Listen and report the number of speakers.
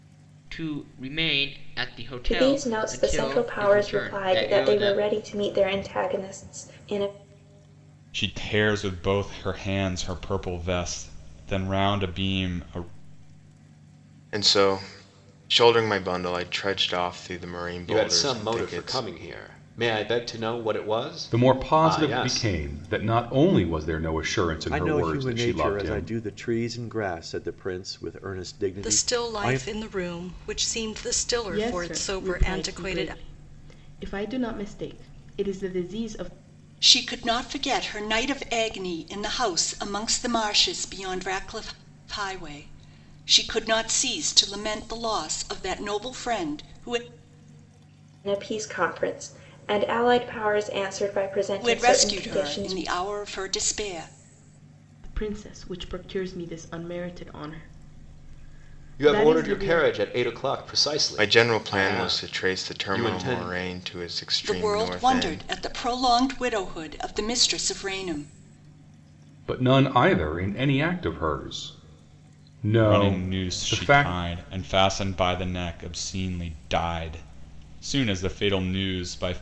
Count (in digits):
10